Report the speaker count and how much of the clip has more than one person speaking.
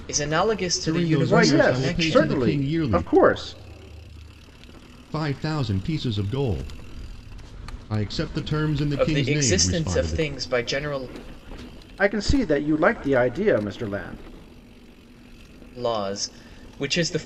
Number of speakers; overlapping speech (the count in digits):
3, about 21%